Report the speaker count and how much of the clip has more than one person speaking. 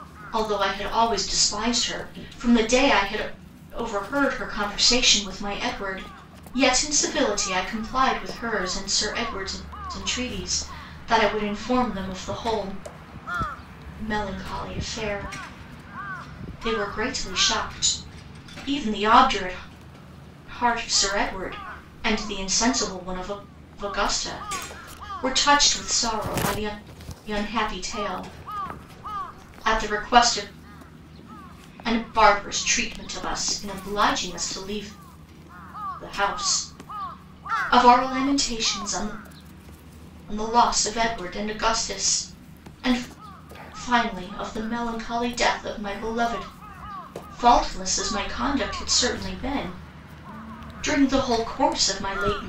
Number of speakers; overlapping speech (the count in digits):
1, no overlap